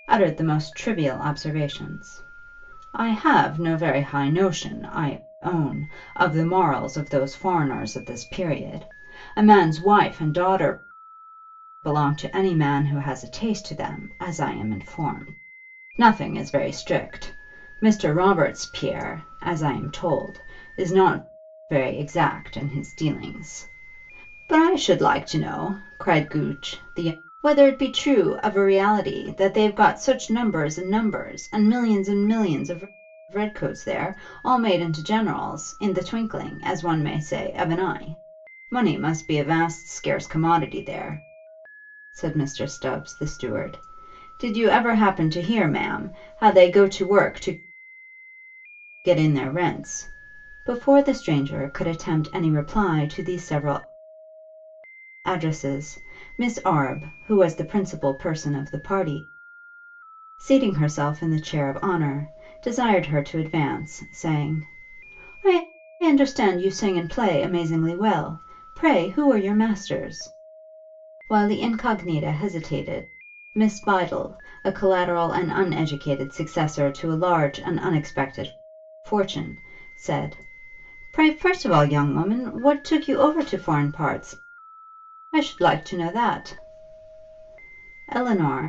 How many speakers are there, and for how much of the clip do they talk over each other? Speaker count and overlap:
one, no overlap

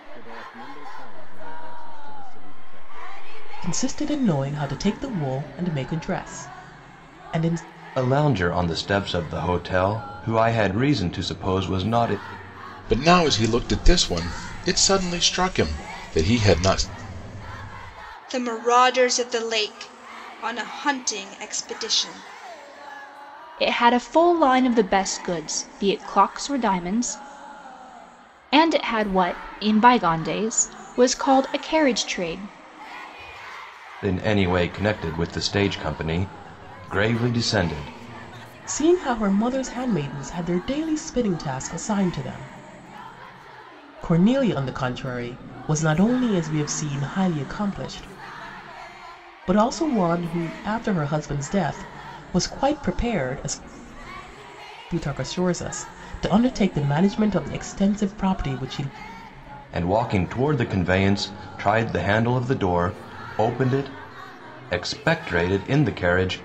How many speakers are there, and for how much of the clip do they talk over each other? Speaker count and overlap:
six, no overlap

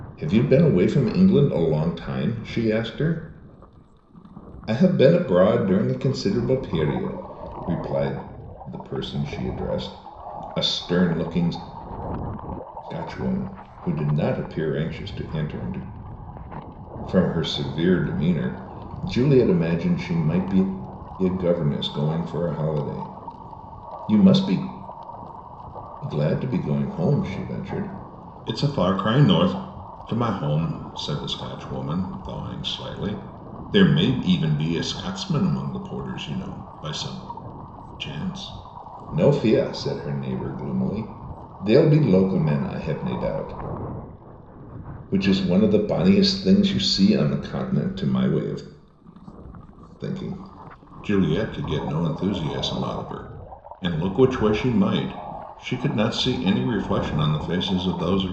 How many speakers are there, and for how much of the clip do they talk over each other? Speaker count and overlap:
one, no overlap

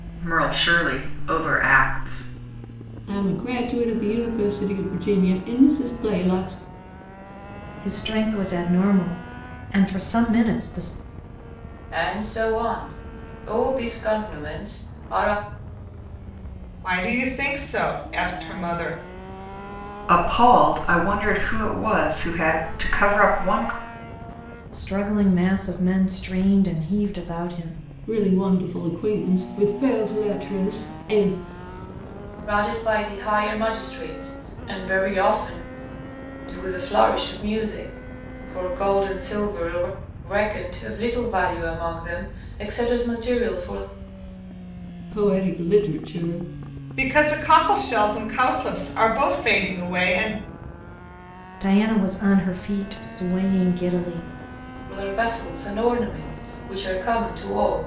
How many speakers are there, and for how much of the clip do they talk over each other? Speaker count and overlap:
five, no overlap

